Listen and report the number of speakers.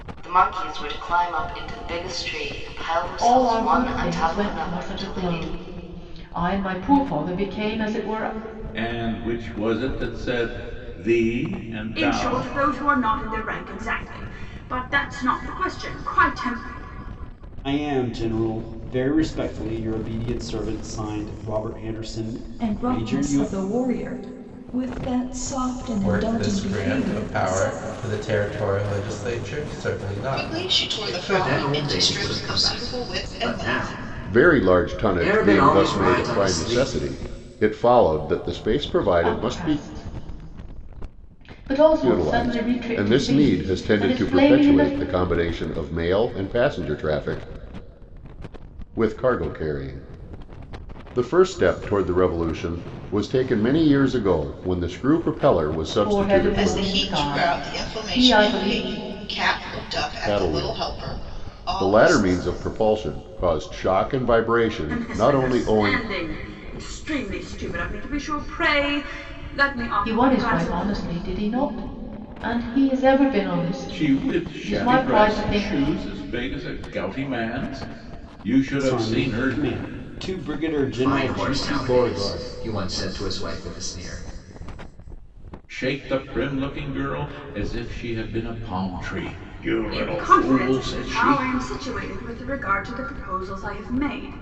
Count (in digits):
10